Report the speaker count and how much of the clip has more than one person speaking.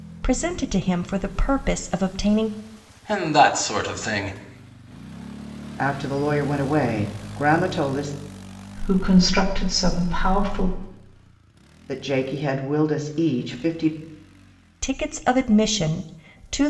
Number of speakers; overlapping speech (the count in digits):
4, no overlap